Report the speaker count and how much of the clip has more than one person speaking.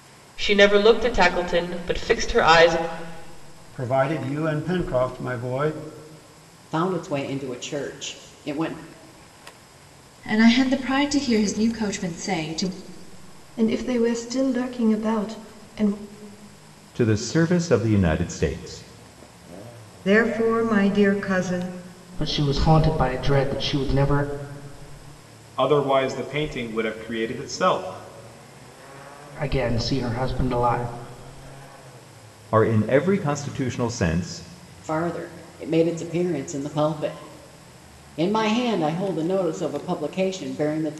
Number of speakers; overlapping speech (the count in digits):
9, no overlap